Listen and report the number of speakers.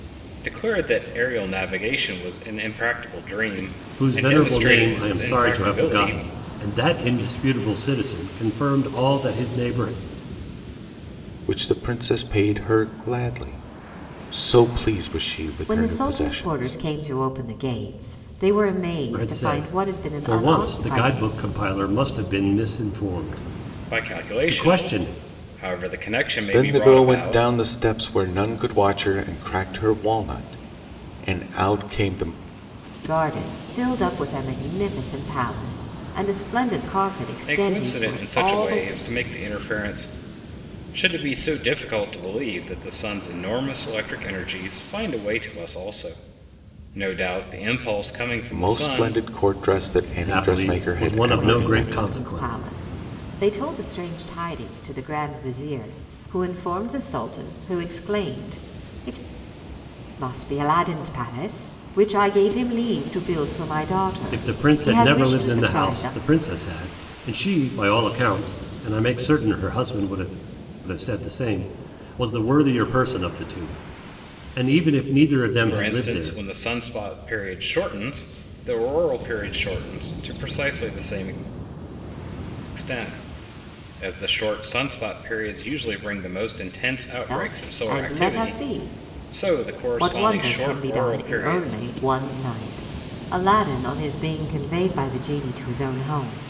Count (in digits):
4